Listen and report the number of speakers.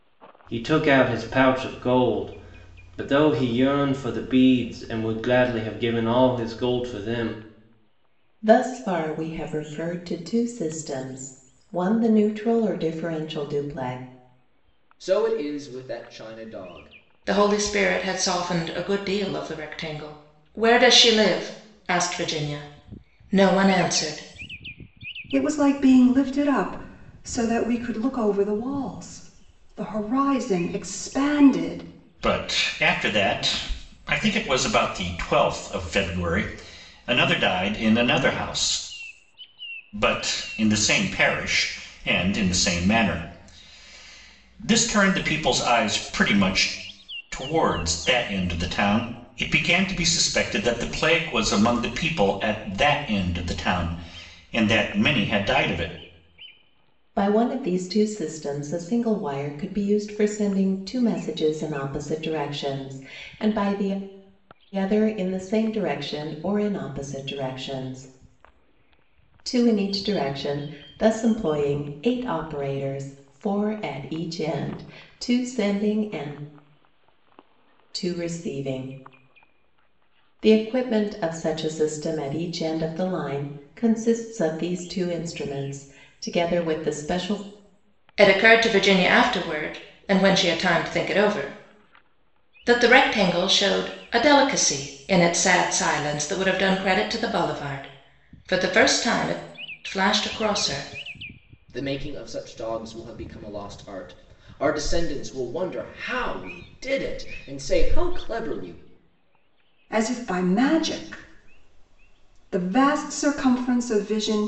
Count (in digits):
6